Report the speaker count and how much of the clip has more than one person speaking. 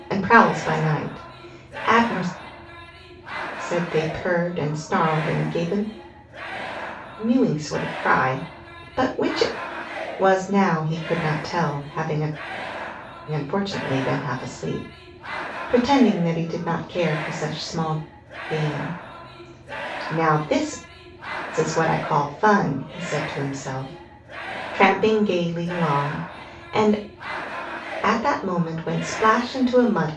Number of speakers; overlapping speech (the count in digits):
1, no overlap